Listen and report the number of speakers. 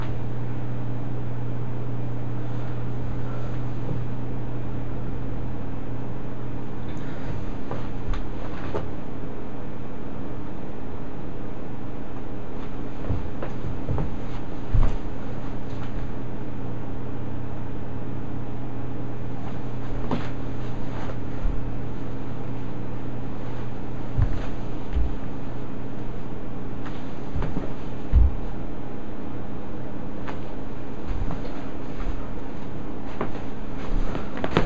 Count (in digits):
0